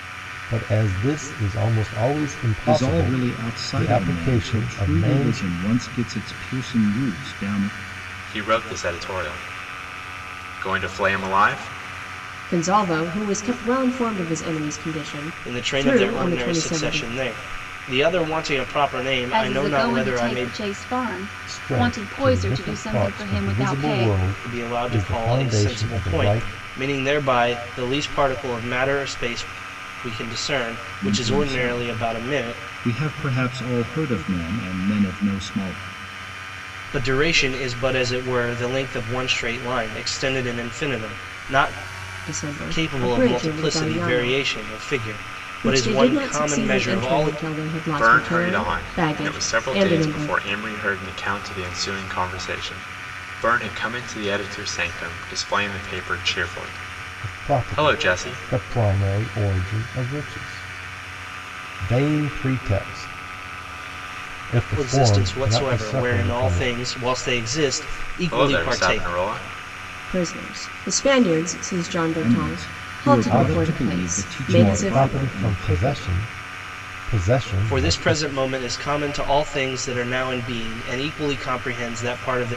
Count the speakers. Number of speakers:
6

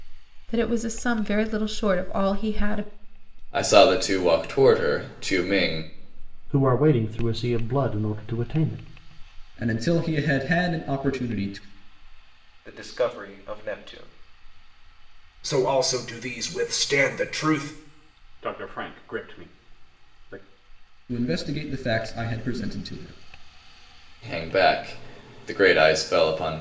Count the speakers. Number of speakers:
7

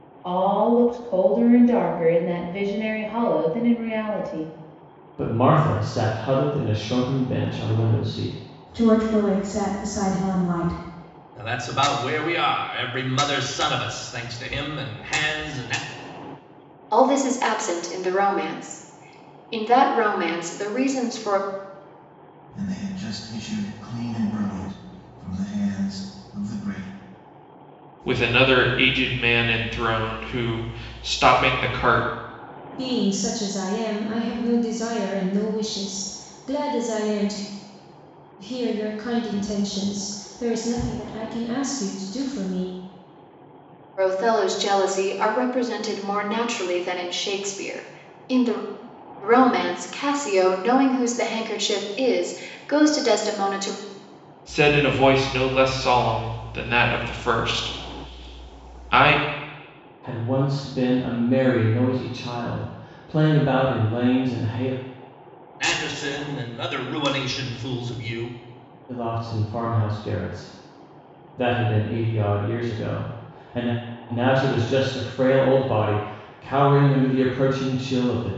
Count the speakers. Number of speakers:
8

